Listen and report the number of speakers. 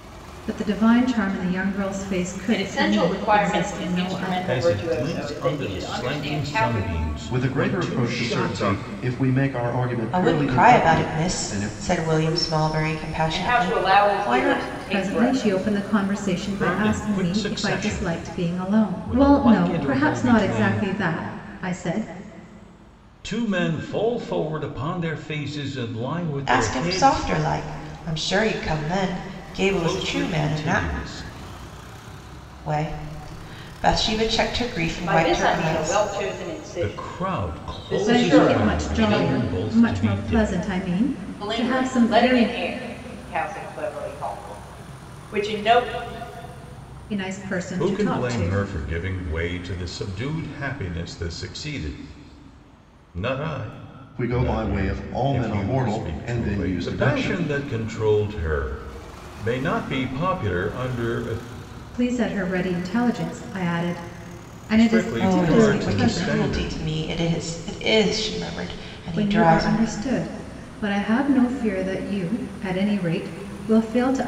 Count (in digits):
5